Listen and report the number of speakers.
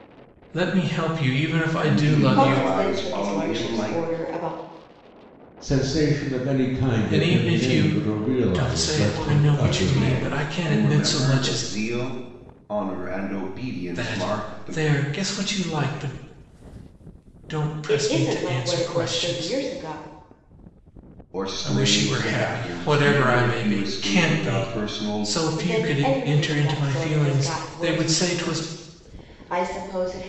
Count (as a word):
four